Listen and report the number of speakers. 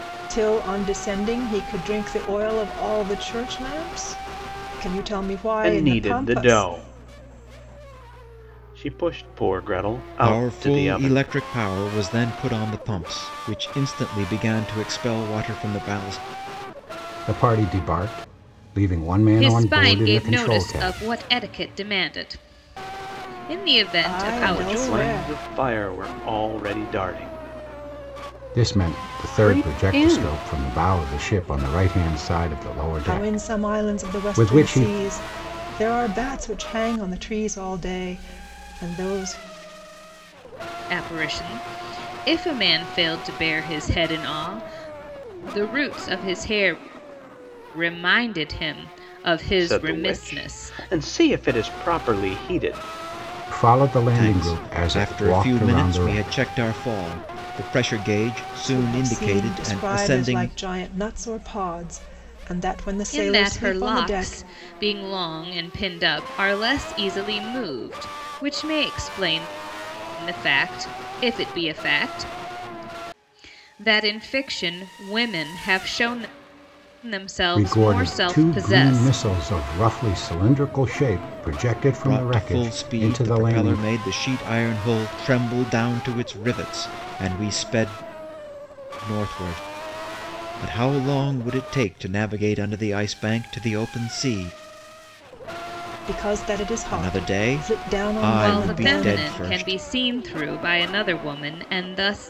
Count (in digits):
5